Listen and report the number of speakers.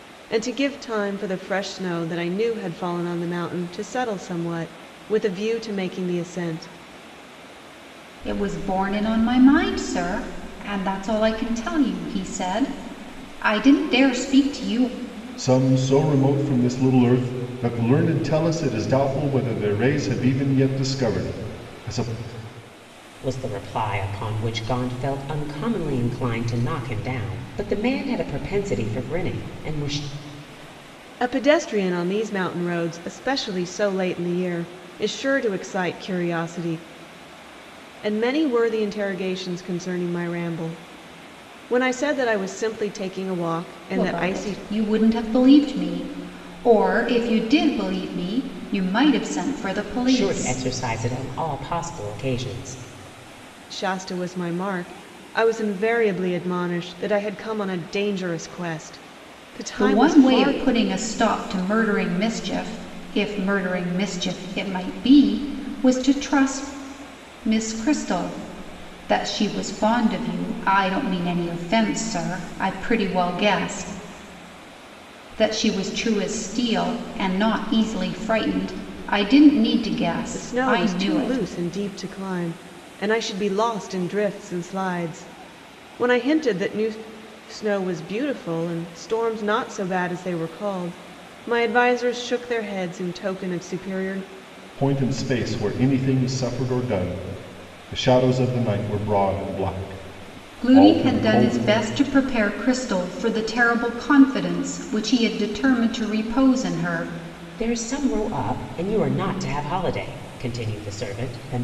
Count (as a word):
four